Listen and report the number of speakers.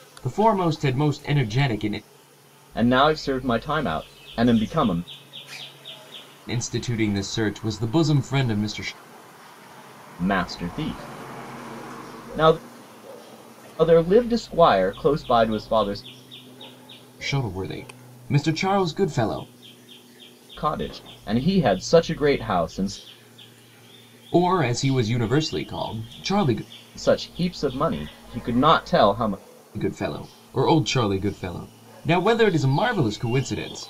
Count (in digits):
2